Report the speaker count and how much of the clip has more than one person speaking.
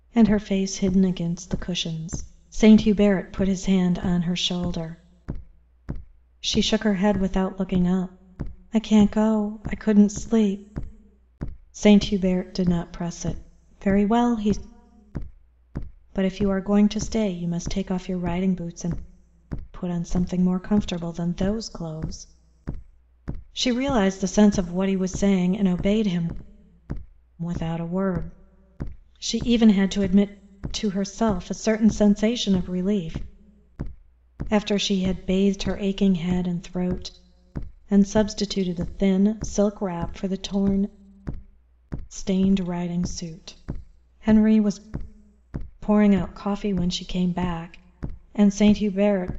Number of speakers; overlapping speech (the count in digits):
1, no overlap